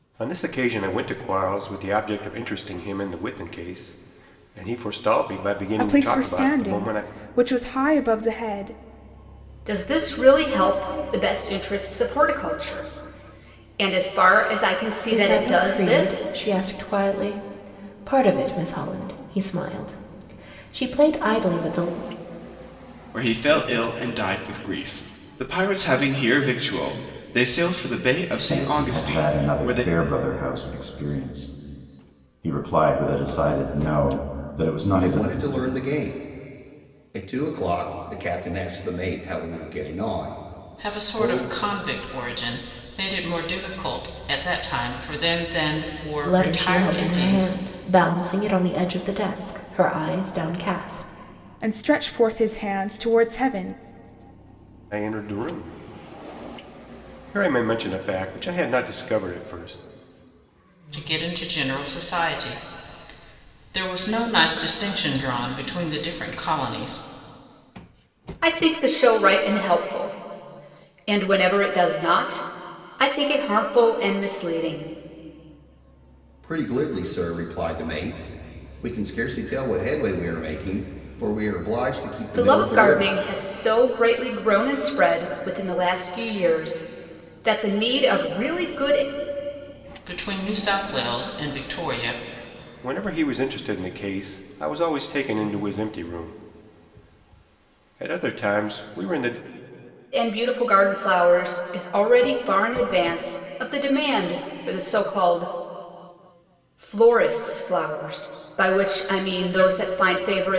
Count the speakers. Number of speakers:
8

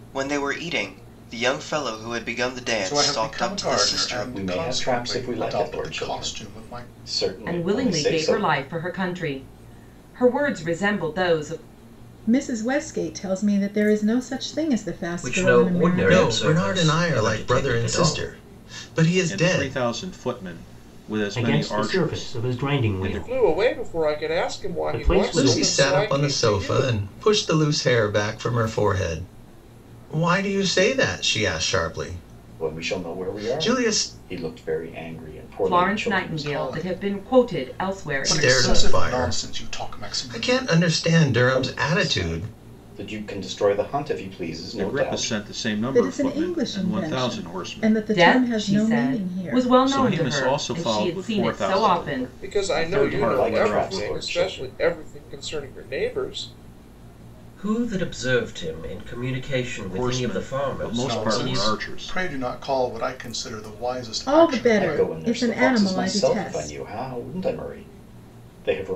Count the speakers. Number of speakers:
10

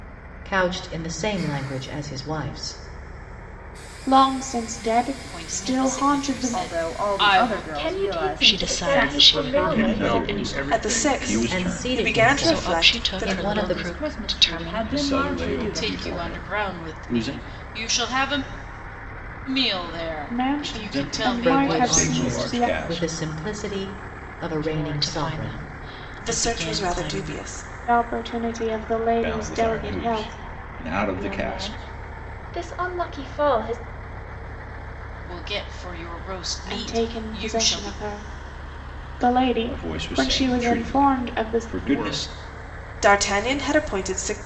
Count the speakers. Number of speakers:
9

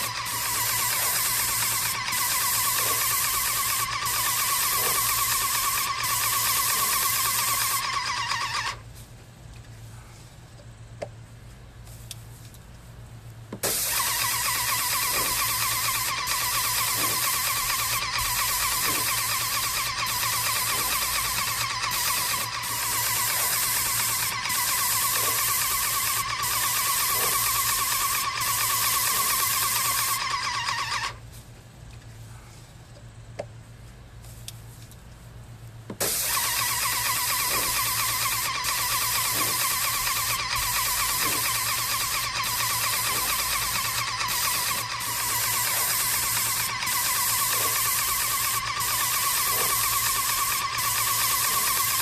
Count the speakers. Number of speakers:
0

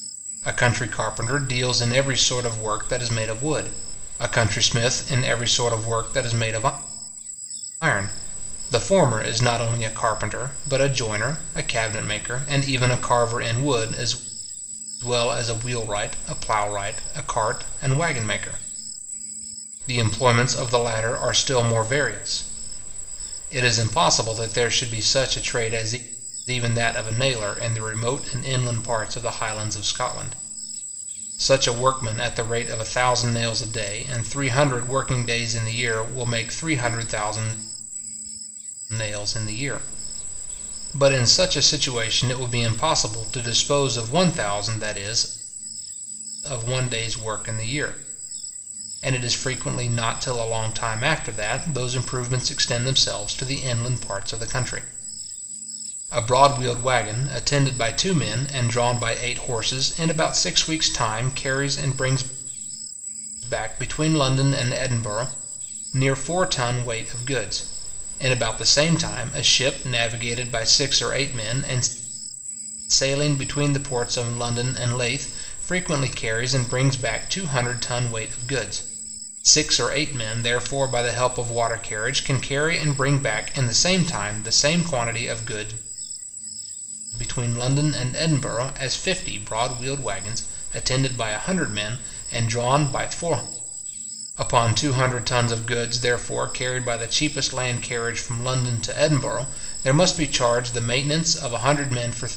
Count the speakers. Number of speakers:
1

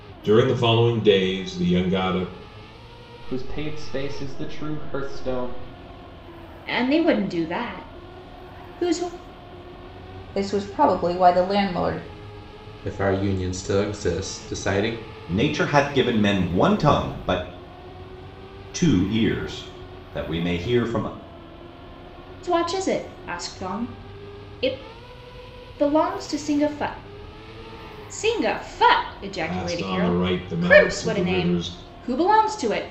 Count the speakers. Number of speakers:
6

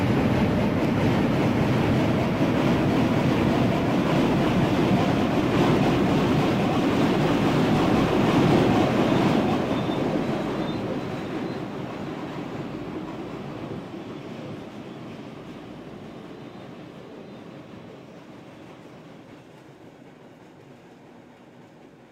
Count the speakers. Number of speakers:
0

